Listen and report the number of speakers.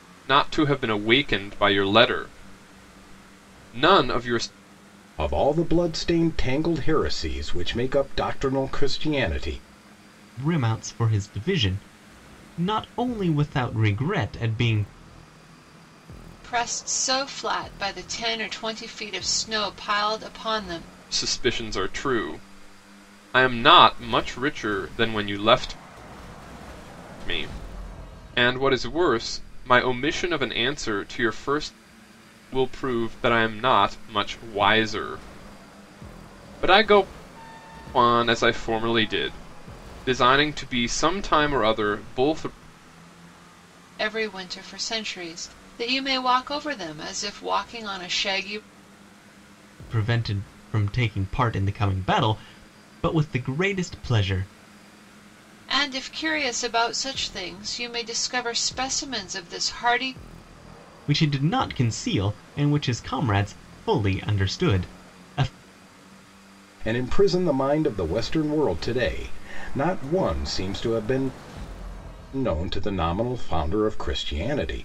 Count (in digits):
4